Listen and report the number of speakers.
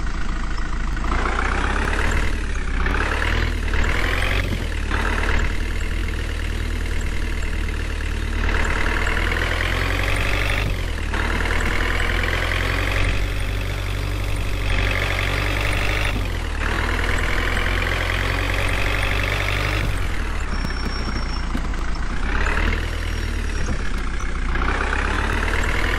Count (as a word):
zero